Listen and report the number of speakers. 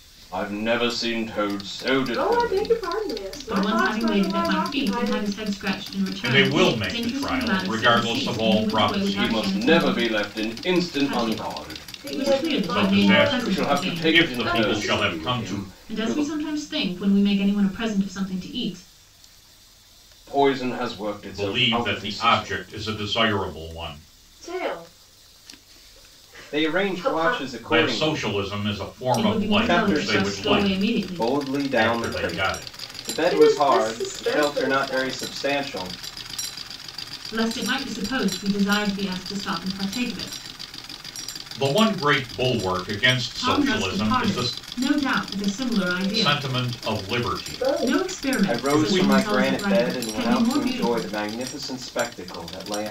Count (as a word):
four